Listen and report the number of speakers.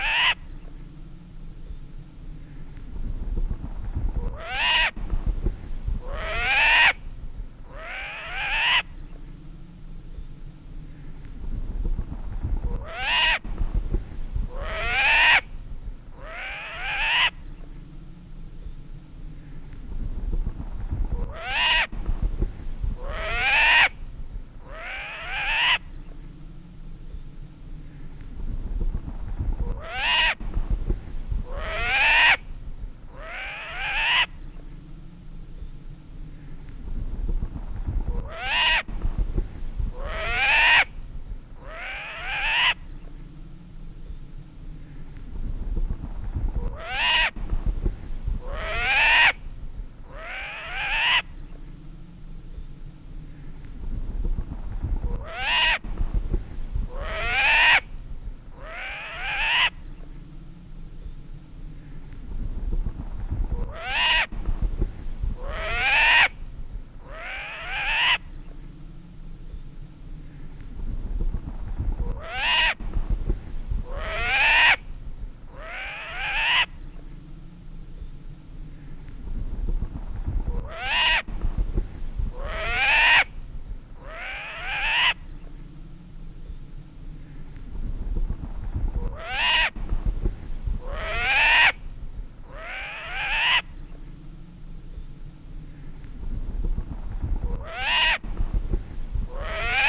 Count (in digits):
0